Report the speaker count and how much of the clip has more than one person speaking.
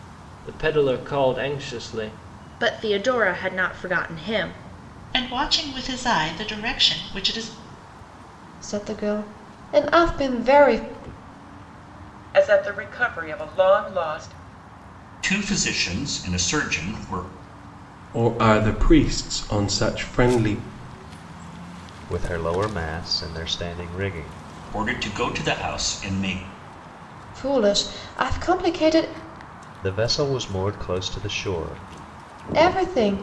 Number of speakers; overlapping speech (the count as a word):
eight, no overlap